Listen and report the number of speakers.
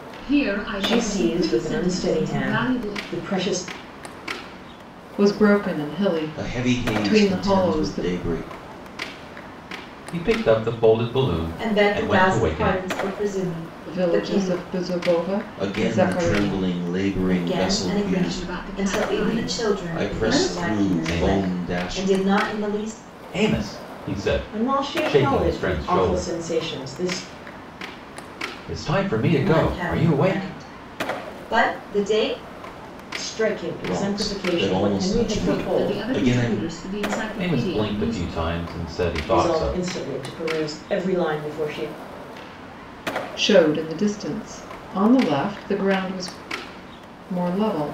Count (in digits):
6